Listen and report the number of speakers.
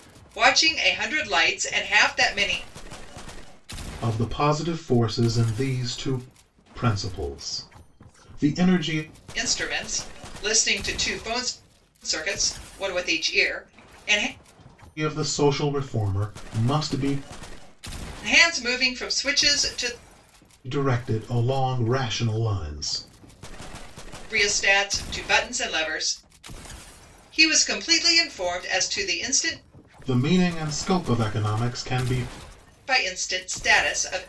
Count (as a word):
two